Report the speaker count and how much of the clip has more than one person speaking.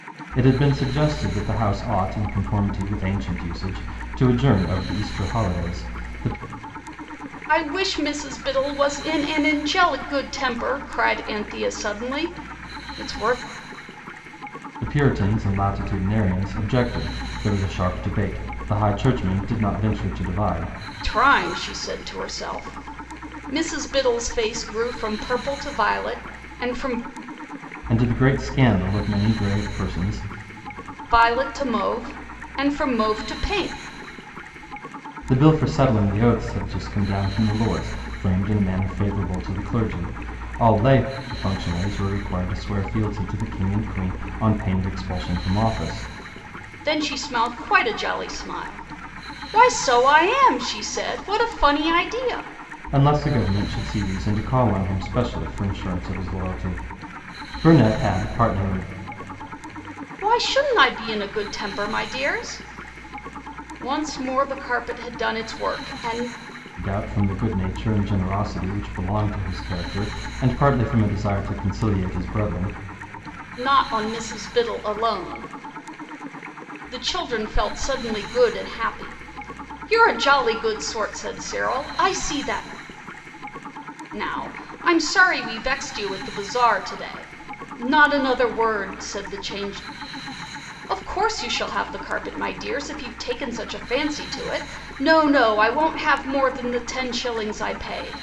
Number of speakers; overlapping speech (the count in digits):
2, no overlap